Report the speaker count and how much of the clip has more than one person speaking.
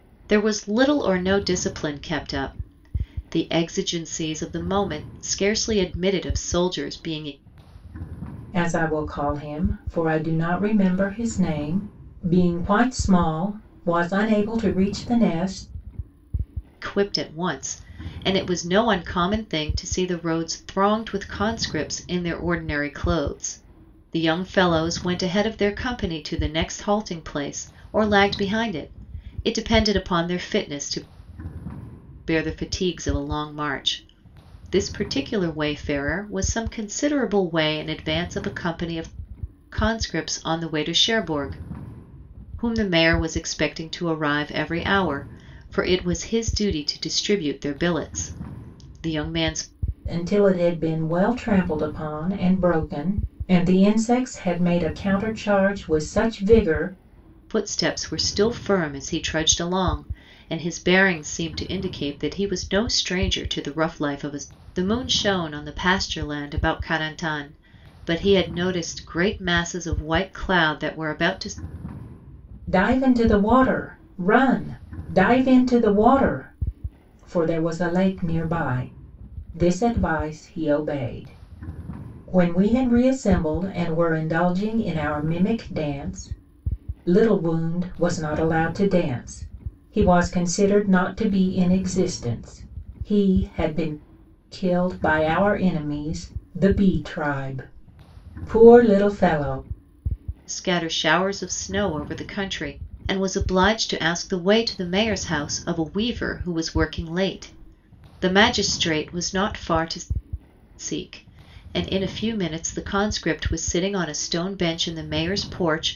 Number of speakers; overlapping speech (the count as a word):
two, no overlap